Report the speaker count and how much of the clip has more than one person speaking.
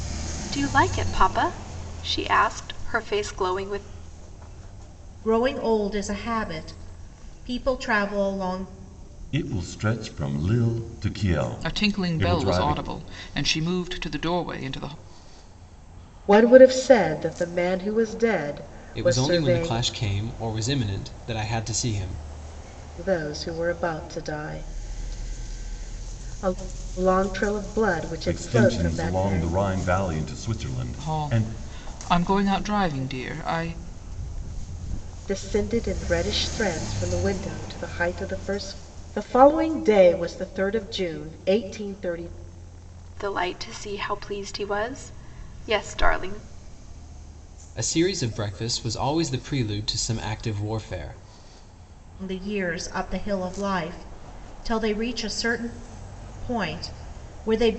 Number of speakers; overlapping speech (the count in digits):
6, about 7%